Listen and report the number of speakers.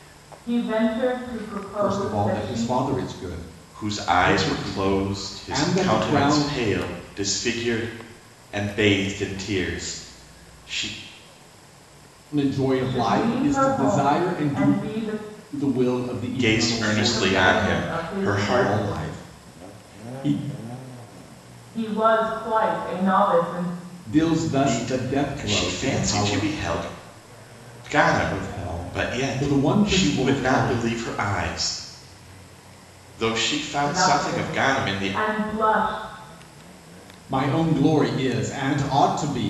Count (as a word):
three